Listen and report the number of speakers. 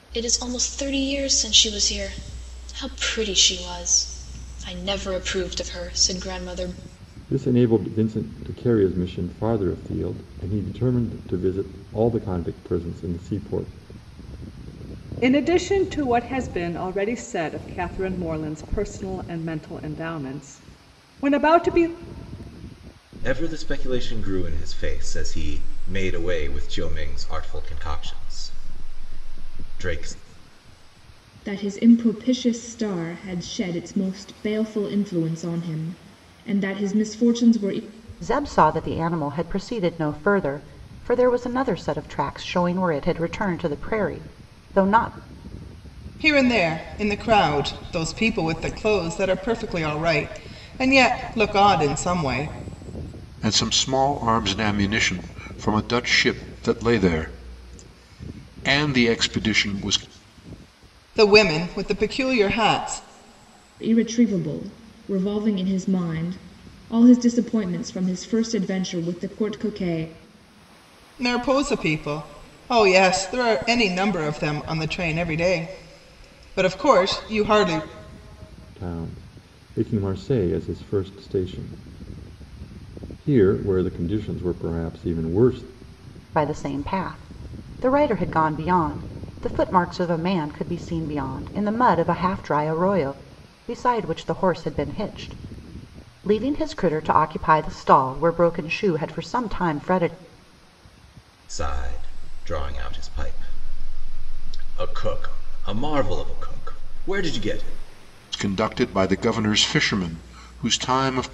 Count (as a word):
eight